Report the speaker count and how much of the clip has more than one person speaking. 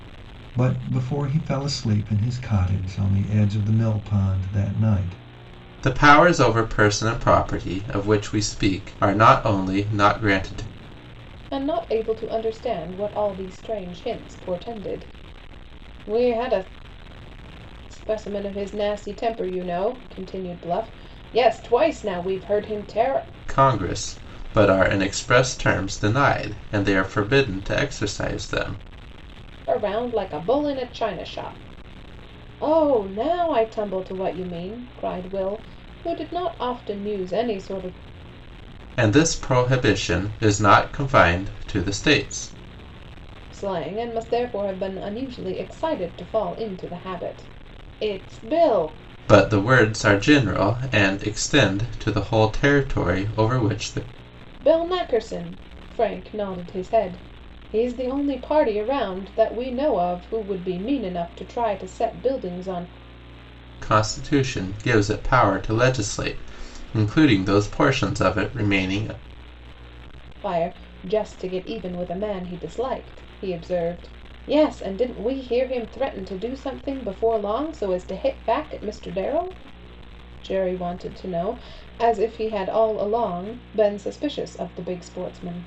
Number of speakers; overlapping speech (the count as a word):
three, no overlap